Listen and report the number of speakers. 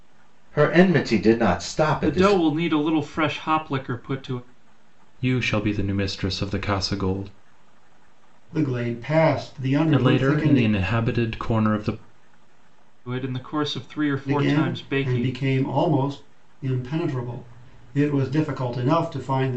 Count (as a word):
four